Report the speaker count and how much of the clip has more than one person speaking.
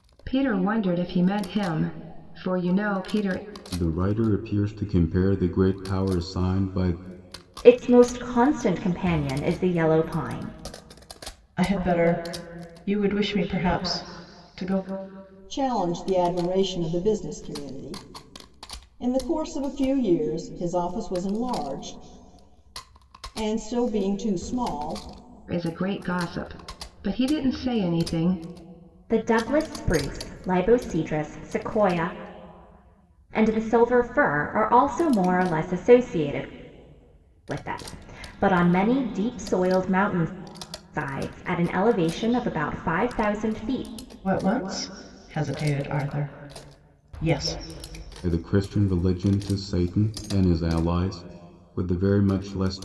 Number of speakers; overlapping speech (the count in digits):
5, no overlap